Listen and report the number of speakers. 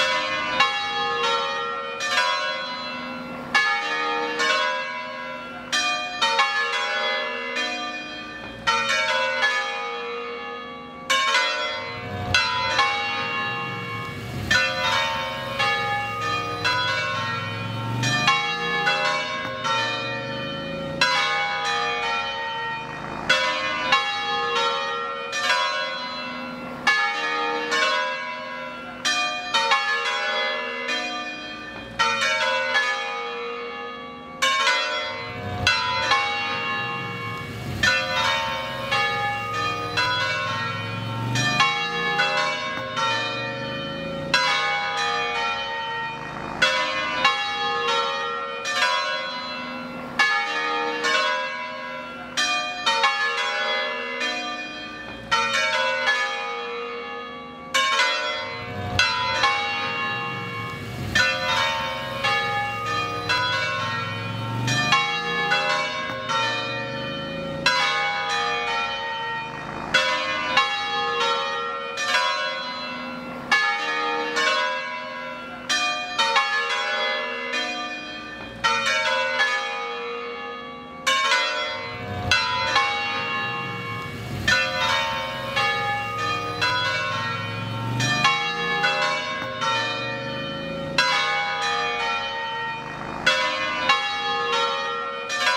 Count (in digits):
0